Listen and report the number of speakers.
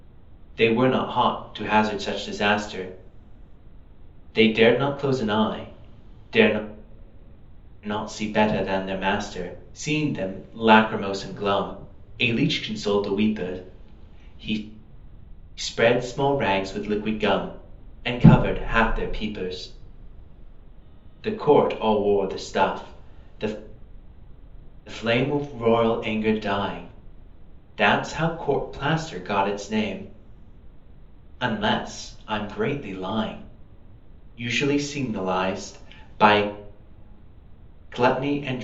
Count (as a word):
one